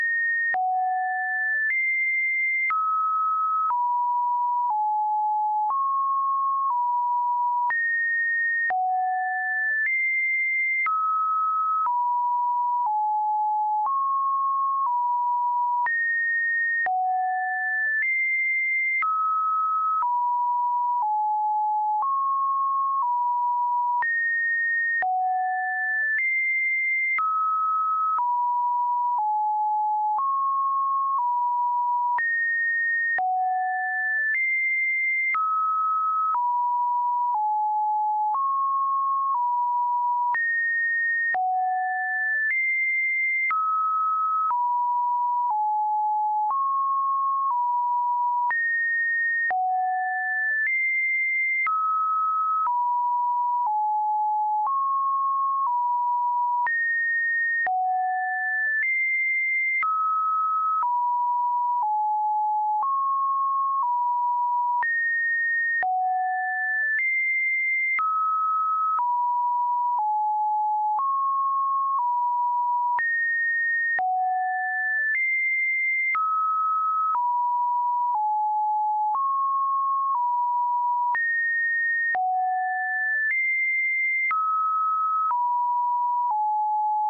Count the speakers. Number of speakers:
0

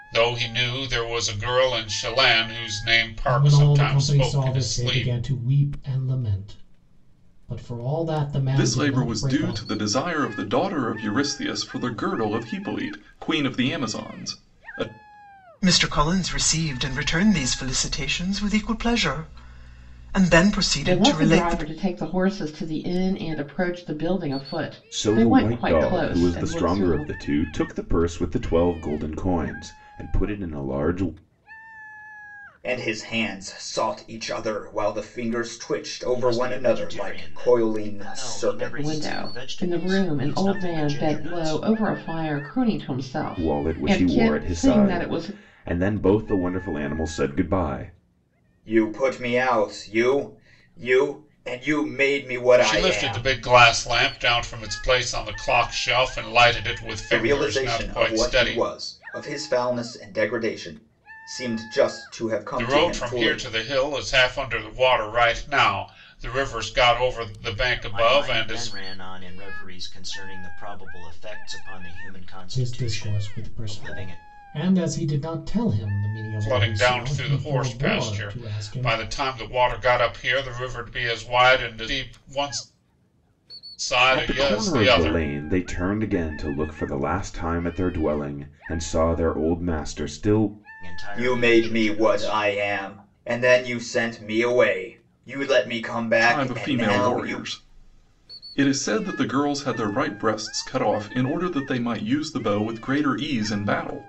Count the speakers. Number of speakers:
8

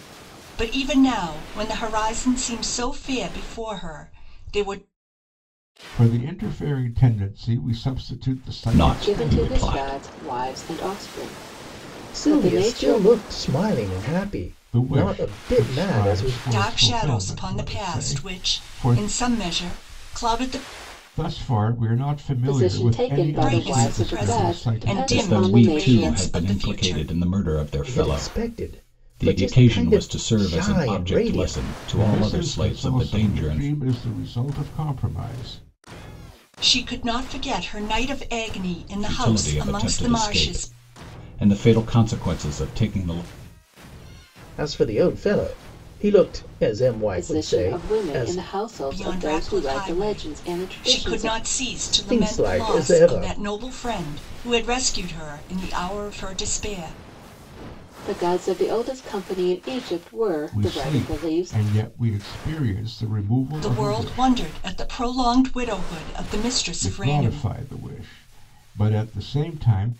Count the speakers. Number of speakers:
5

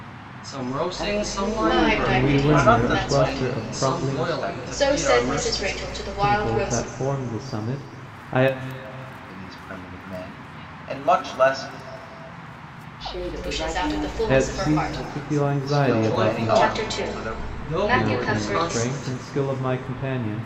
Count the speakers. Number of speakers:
5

